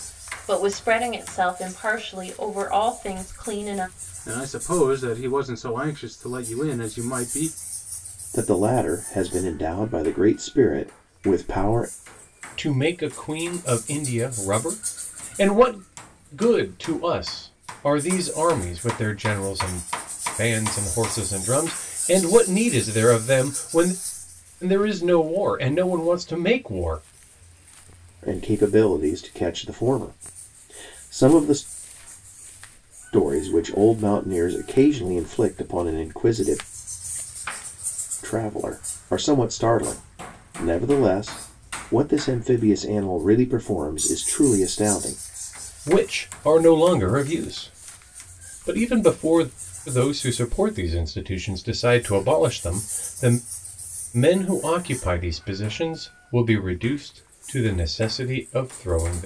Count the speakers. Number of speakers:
four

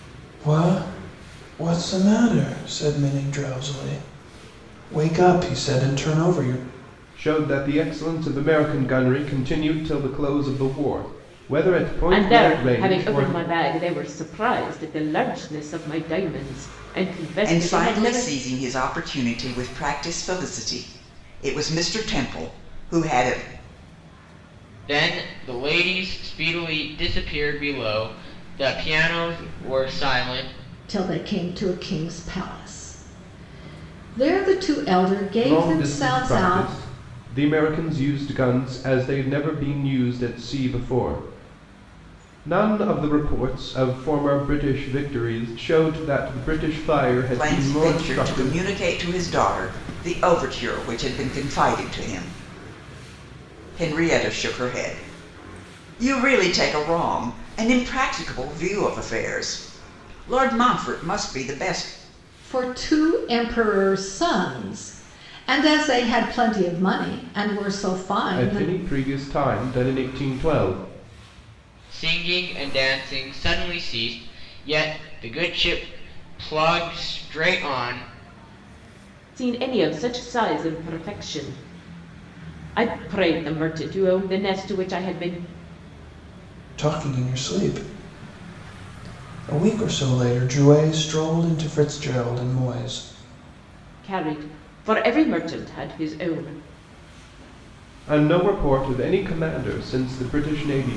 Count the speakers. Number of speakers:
six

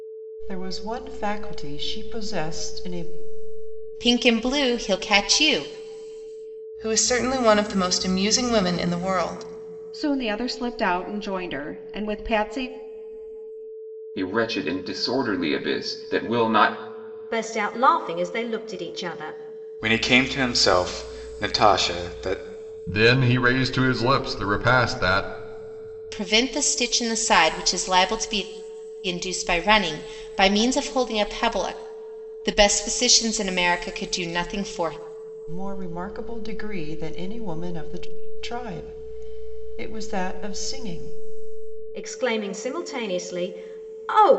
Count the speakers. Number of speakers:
eight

